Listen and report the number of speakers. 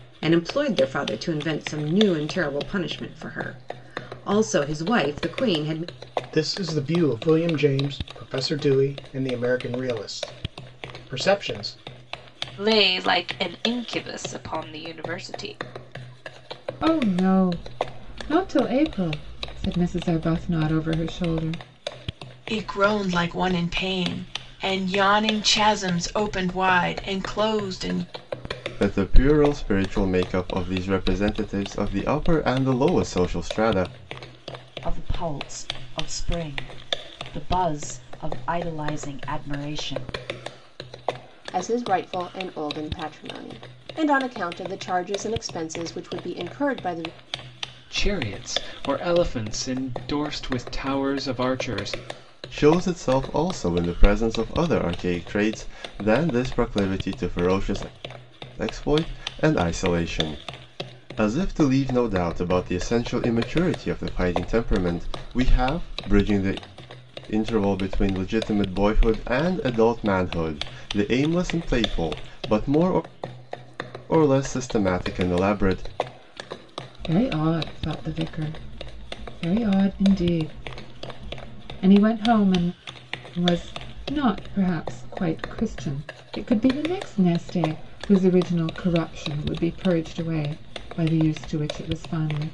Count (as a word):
nine